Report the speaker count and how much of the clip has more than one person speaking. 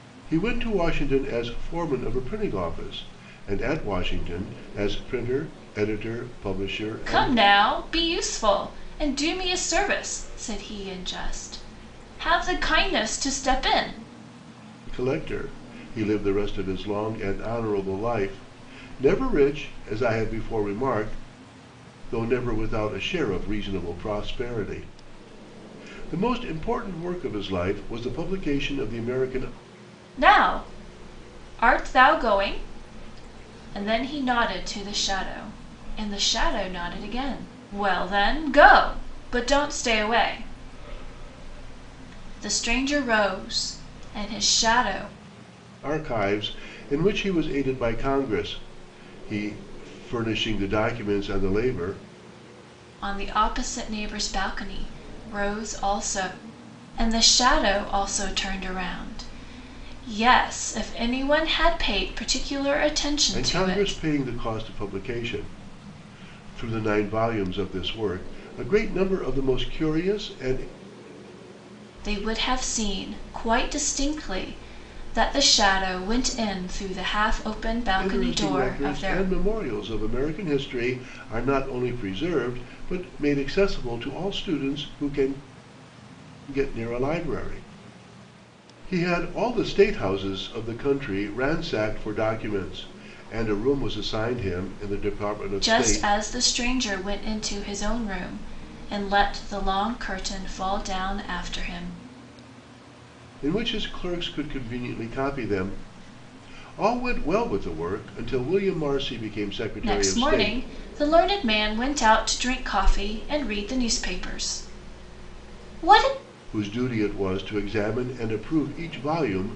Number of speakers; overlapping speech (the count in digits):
2, about 3%